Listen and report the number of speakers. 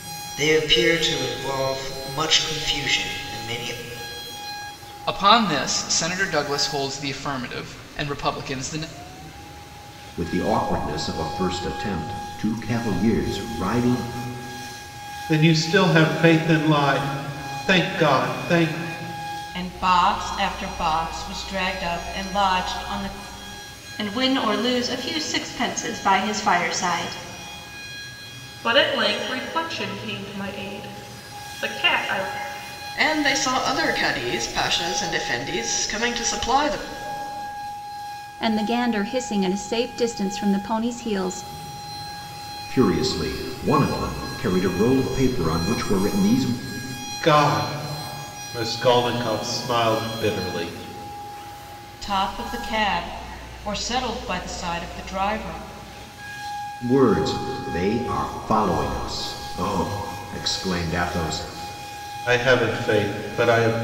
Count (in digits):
9